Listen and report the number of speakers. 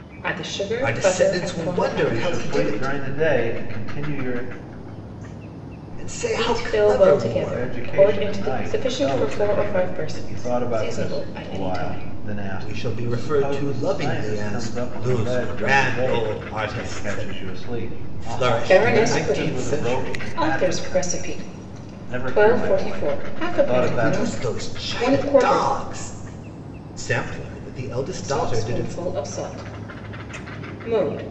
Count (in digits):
3